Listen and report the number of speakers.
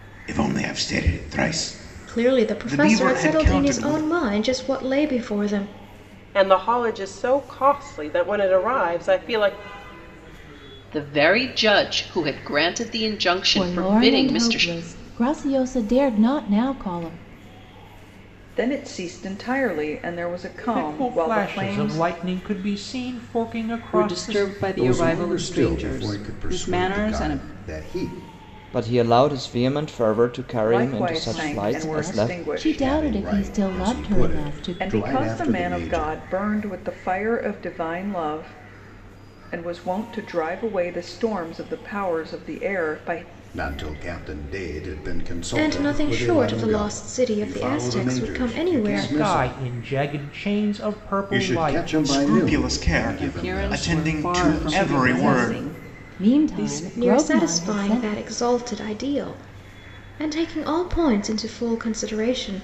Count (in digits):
10